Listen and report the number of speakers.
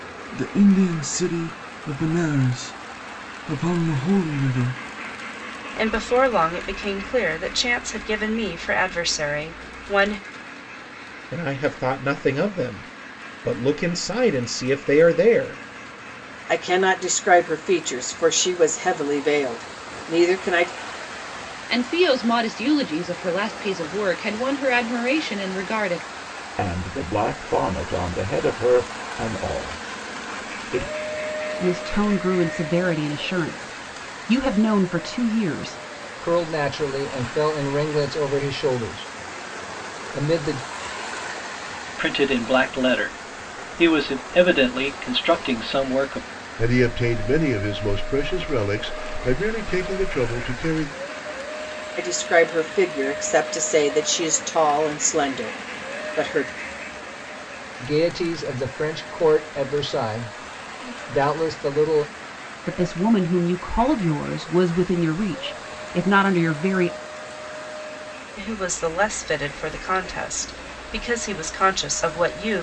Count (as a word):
ten